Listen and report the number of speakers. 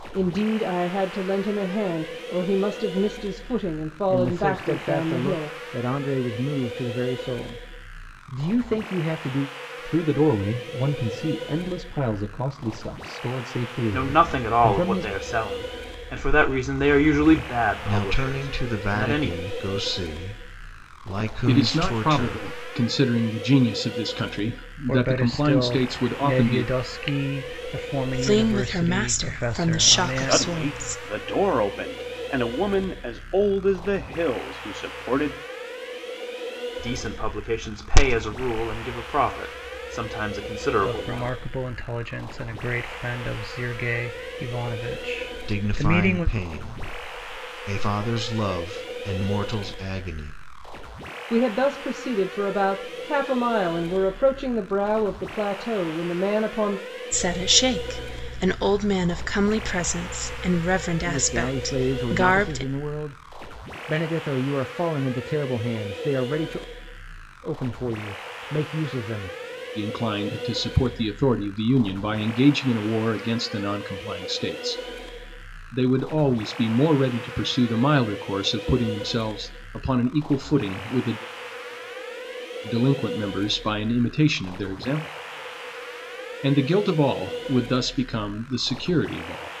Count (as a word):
nine